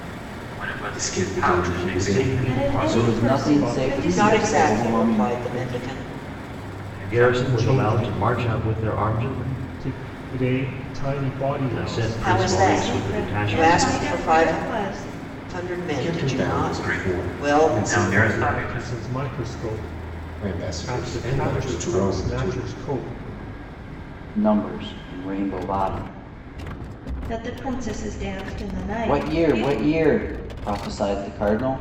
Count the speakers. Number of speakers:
7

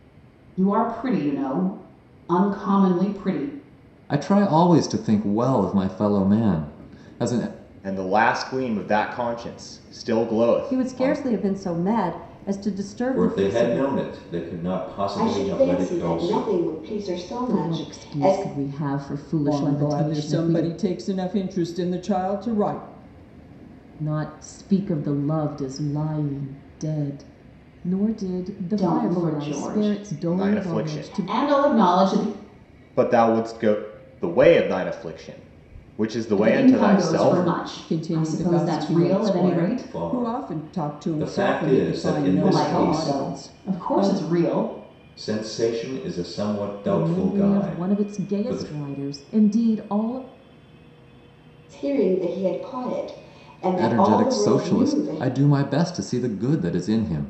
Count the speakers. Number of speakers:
8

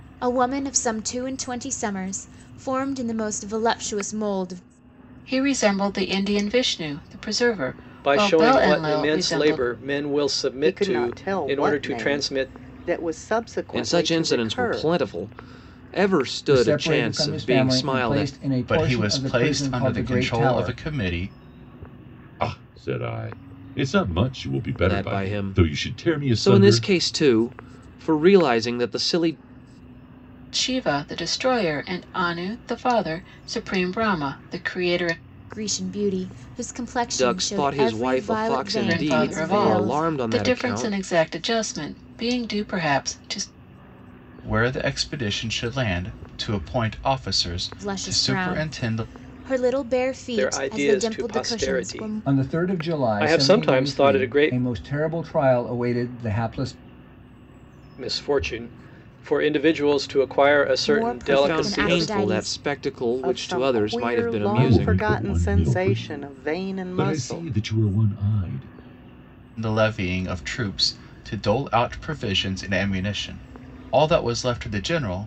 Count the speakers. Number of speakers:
8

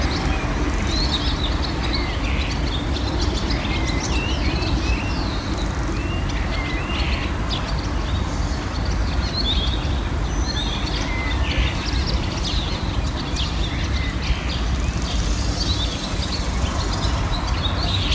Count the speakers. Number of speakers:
0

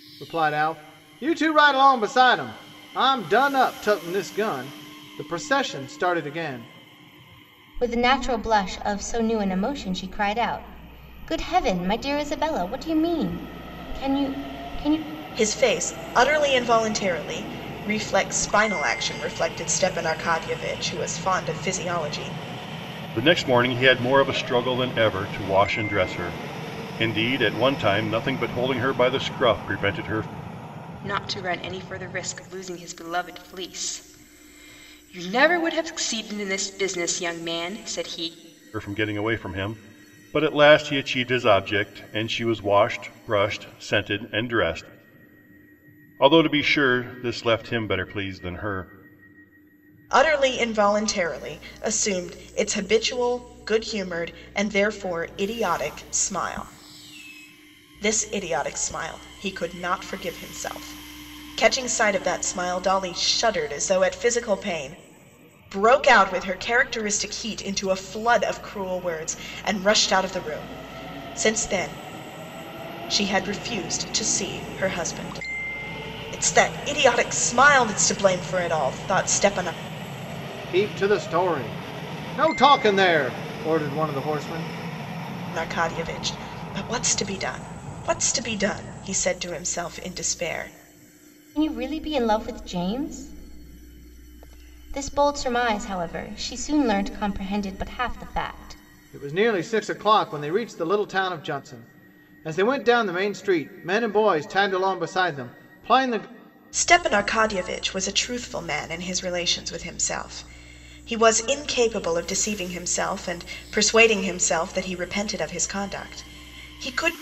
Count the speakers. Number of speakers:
5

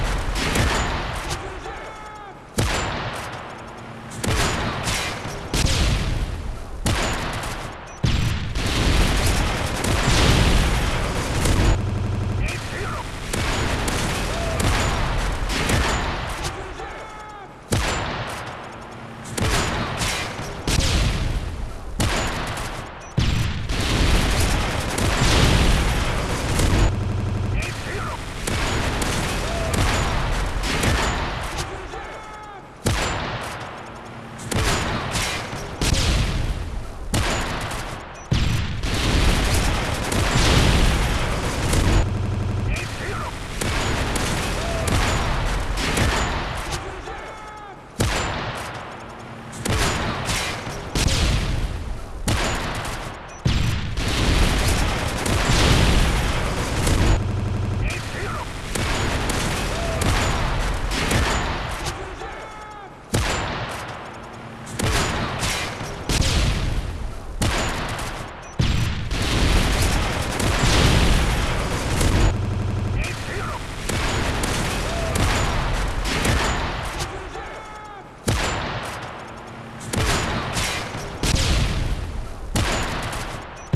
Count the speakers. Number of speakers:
0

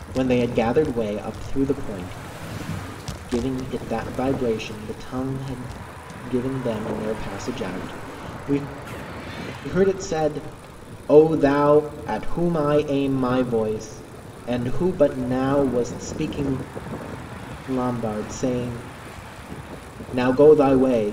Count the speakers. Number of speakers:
1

